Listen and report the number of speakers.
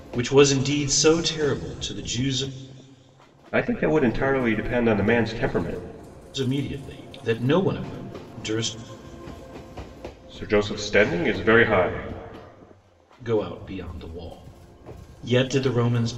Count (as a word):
two